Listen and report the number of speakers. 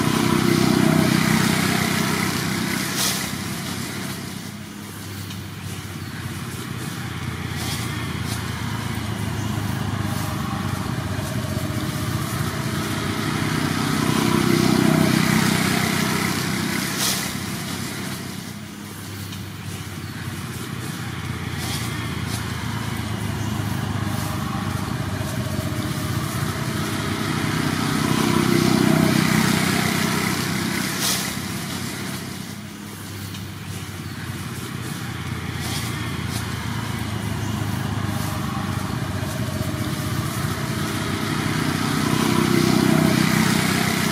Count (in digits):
0